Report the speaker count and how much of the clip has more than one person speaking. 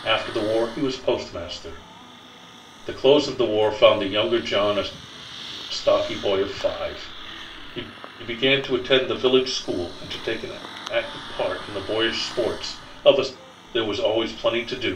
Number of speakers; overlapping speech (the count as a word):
one, no overlap